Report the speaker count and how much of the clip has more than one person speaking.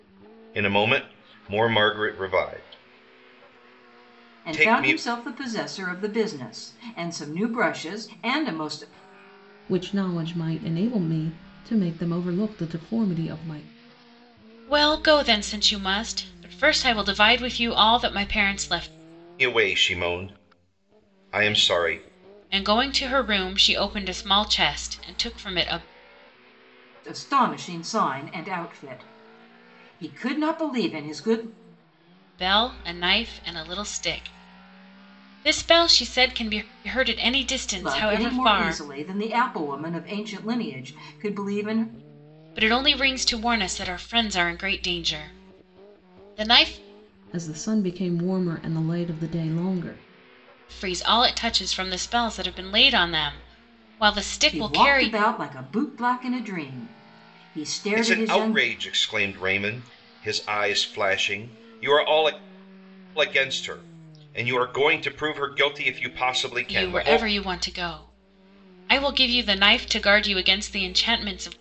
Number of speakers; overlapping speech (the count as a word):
four, about 6%